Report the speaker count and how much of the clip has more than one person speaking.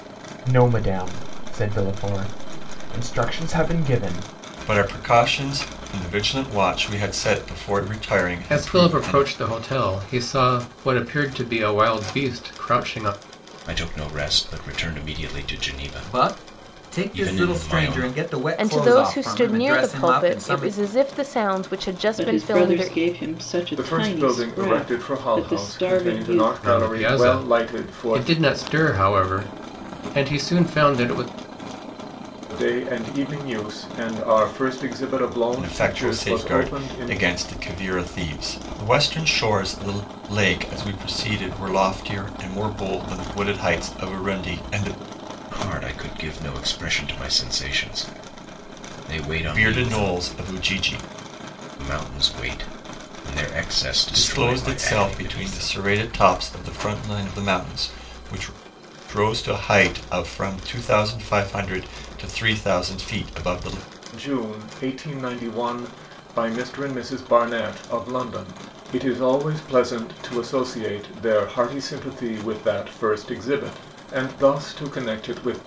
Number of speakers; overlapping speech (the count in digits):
8, about 19%